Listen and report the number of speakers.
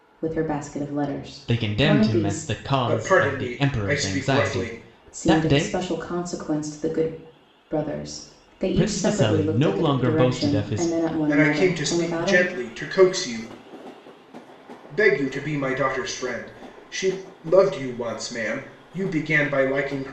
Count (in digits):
3